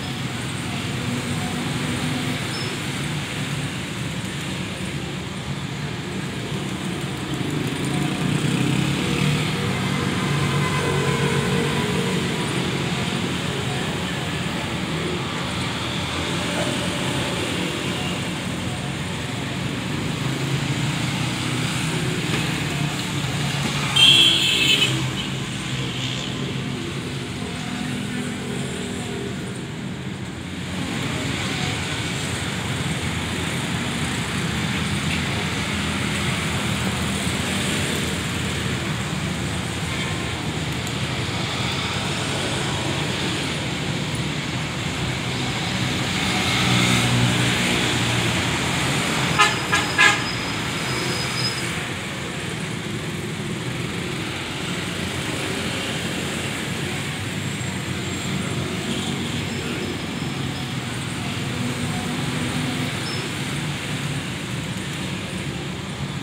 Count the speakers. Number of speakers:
zero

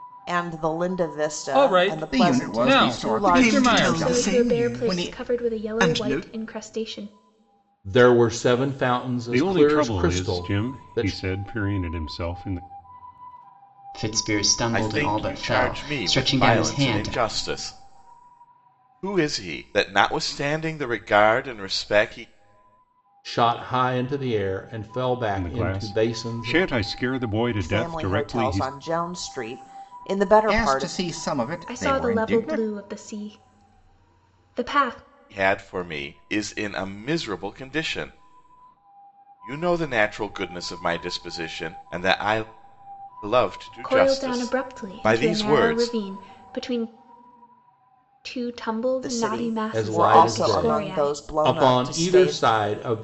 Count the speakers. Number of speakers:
nine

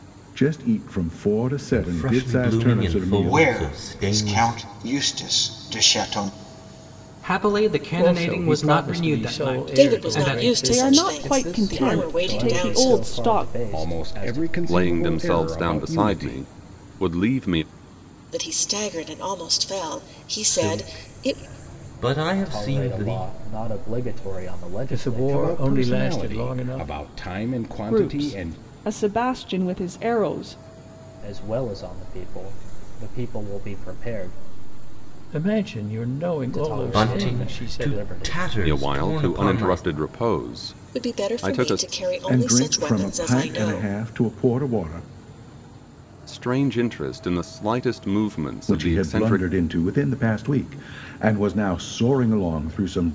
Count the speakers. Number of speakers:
ten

